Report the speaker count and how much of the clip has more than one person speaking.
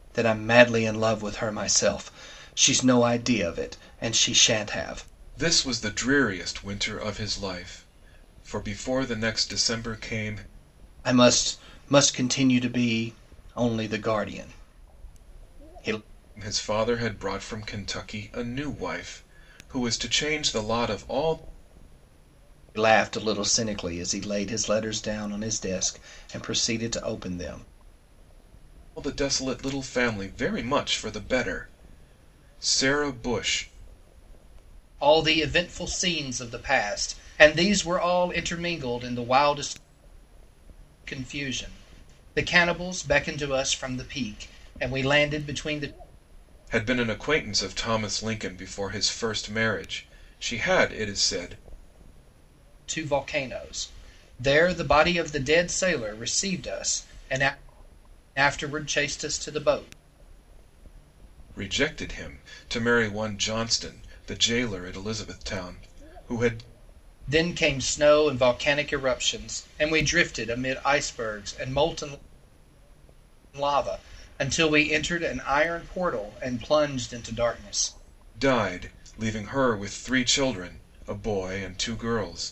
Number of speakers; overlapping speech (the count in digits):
2, no overlap